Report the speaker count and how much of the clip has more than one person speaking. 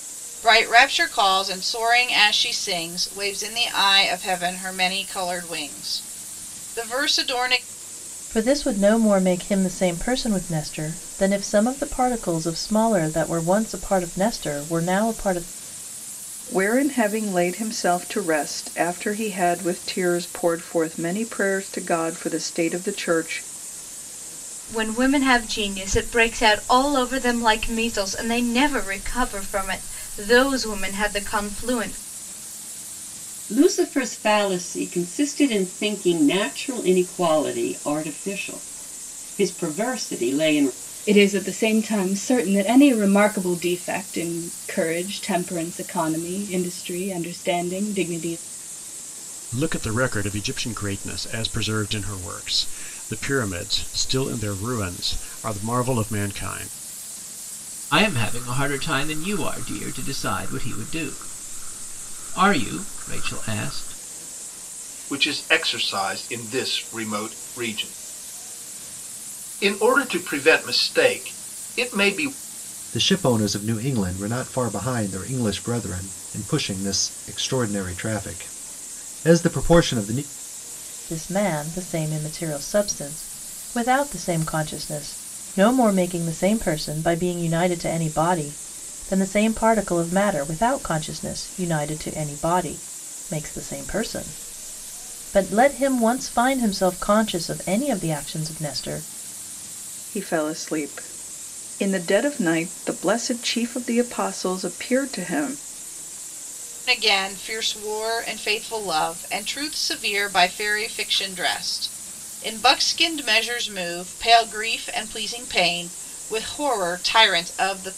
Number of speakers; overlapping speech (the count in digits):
10, no overlap